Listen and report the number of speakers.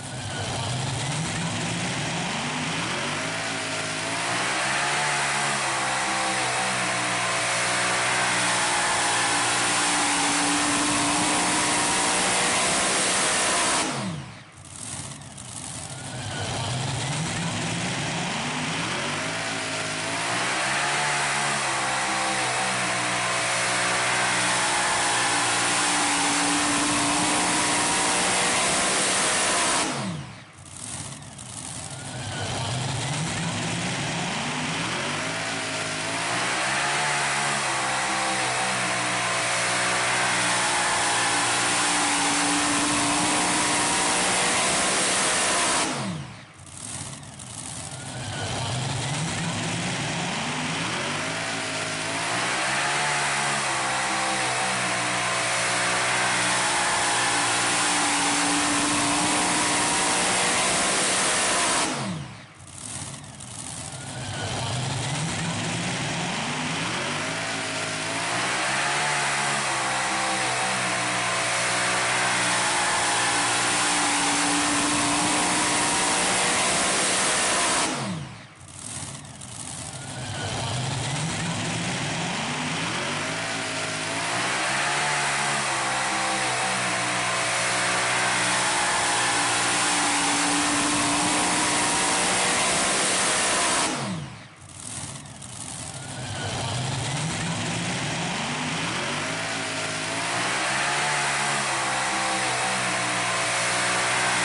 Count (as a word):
zero